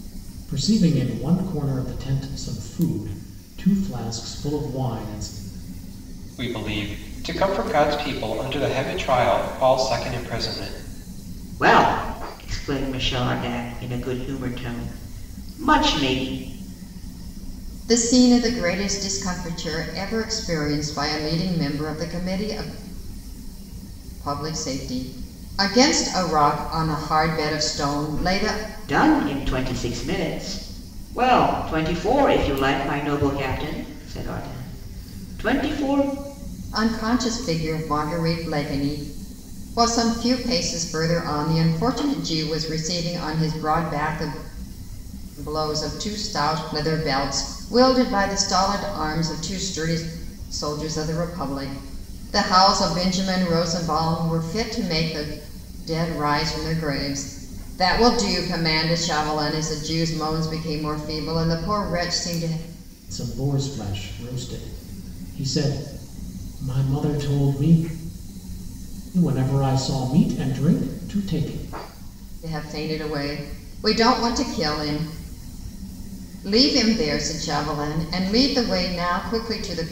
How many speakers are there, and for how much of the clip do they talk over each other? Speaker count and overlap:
four, no overlap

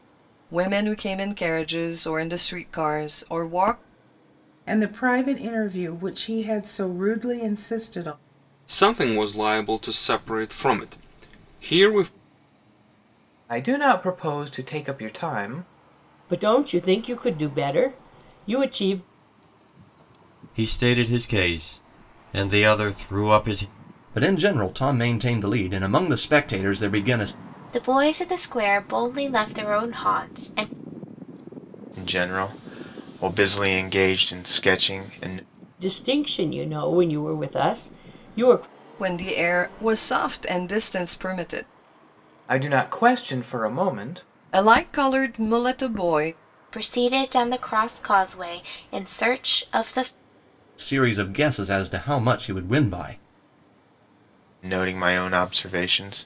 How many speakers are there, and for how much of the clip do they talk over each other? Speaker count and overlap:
nine, no overlap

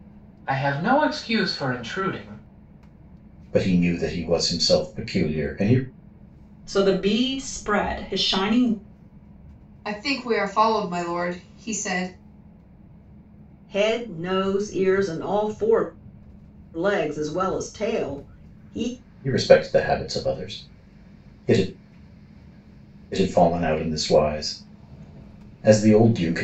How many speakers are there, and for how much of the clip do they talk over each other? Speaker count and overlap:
five, no overlap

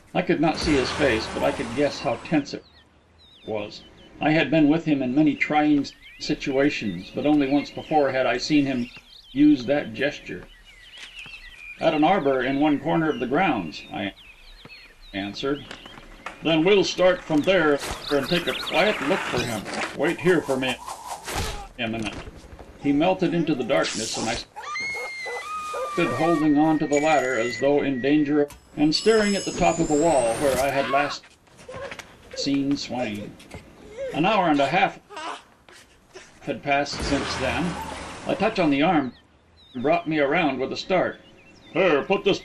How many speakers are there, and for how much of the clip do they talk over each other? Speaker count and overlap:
one, no overlap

